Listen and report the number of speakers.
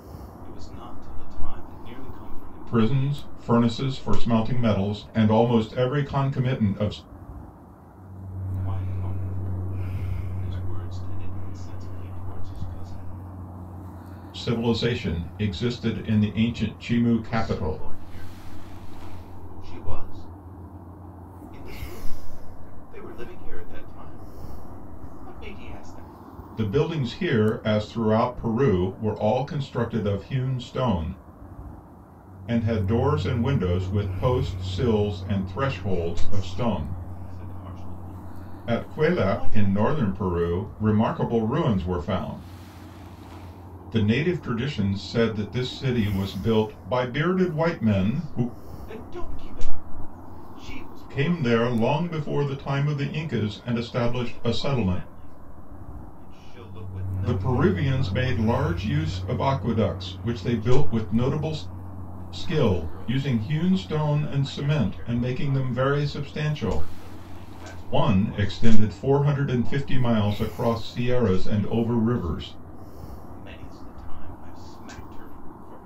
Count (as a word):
two